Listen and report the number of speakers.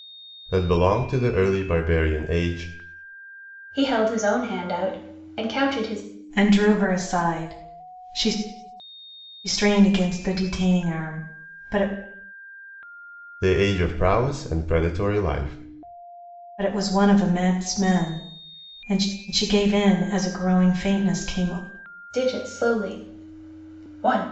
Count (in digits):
3